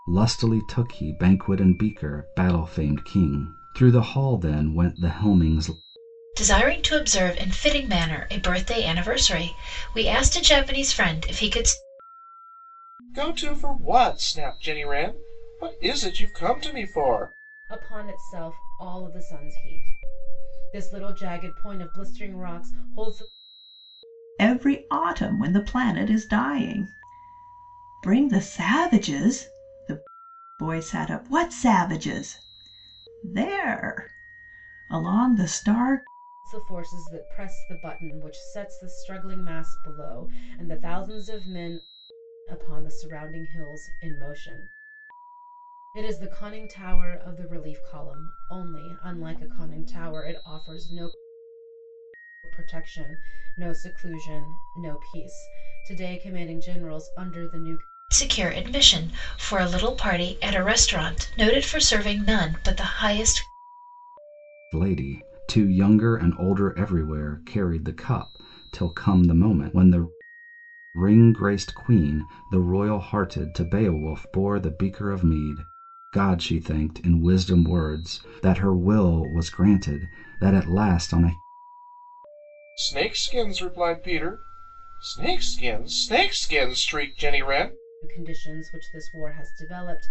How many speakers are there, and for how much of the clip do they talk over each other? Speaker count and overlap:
5, no overlap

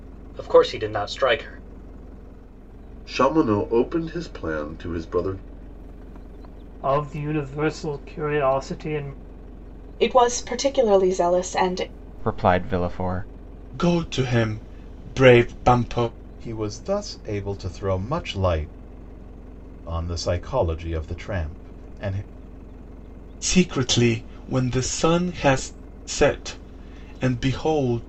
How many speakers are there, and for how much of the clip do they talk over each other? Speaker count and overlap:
7, no overlap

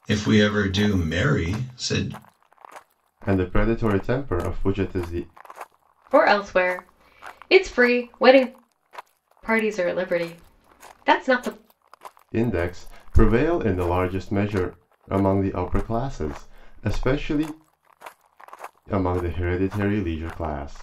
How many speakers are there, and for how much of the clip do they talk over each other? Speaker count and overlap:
3, no overlap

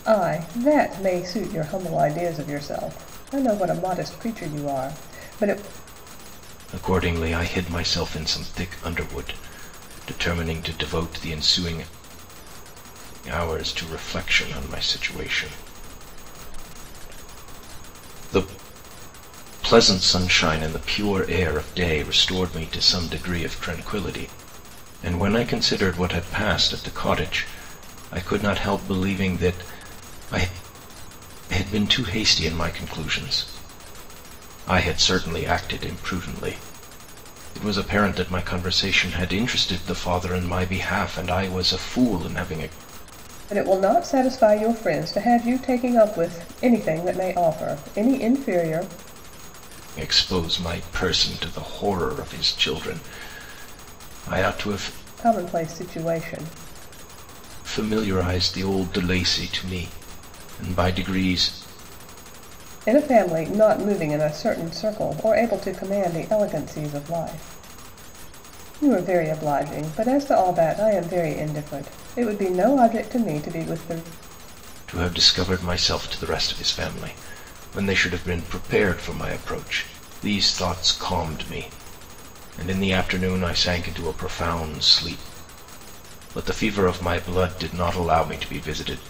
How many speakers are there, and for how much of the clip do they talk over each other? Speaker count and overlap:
2, no overlap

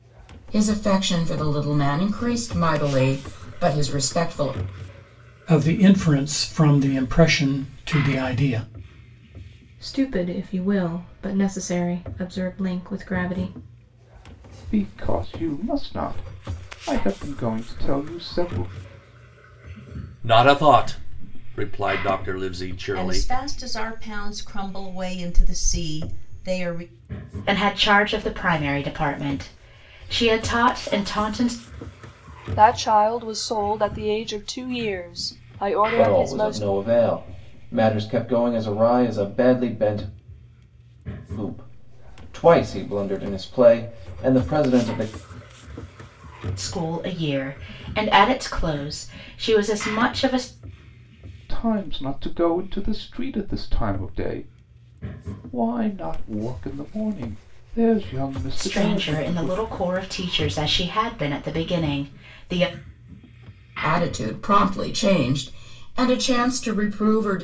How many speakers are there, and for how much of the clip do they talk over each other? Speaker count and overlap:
9, about 3%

